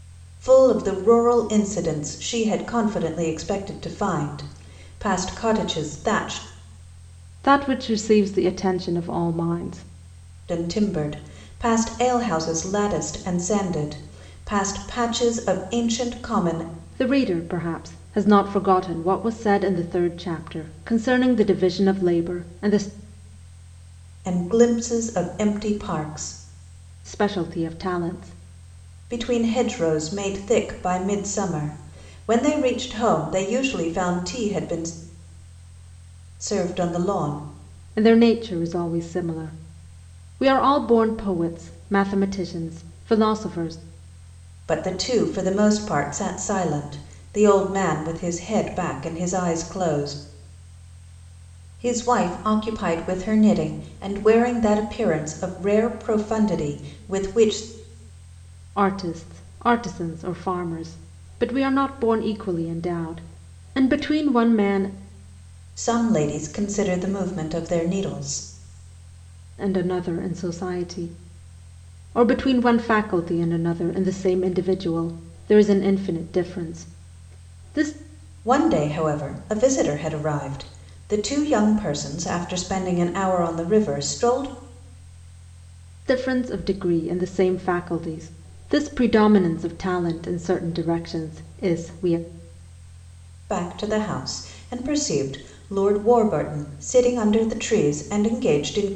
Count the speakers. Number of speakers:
2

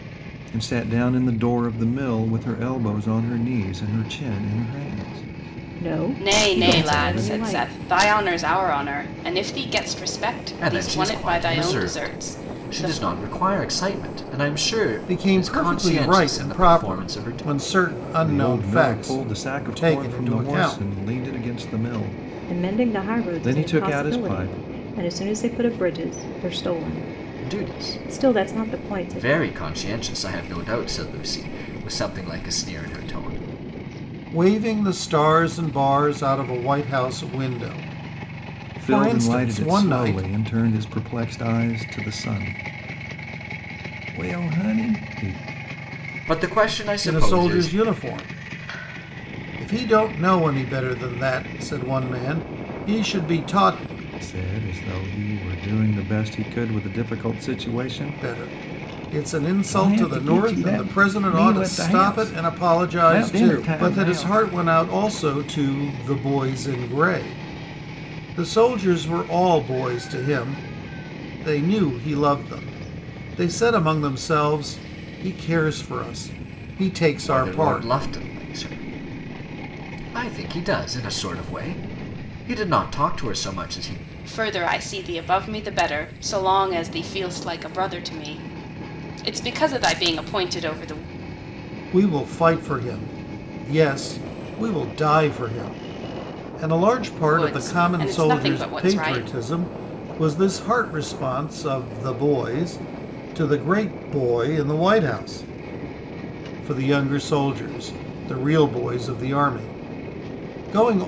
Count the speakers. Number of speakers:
5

